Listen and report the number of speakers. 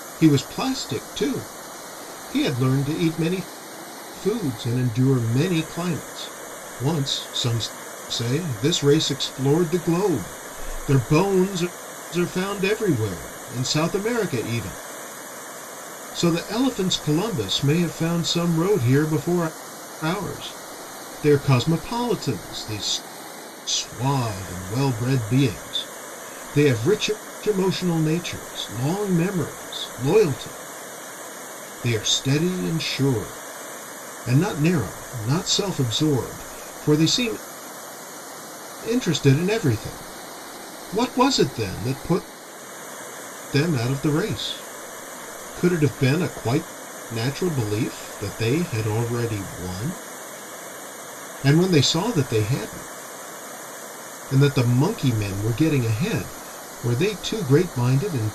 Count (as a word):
one